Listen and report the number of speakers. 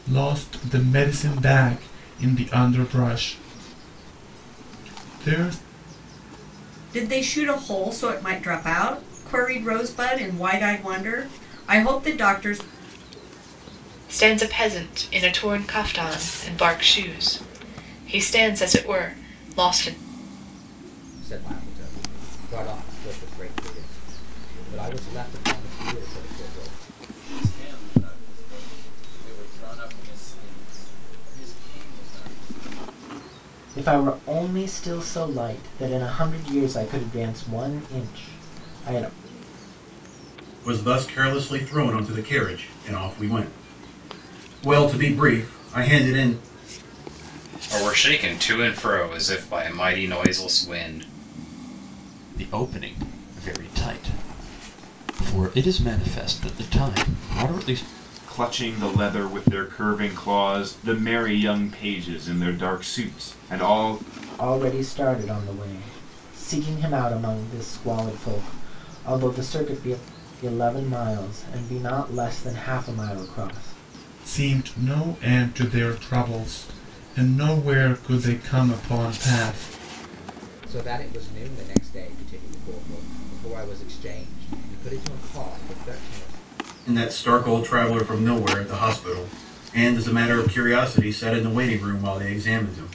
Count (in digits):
10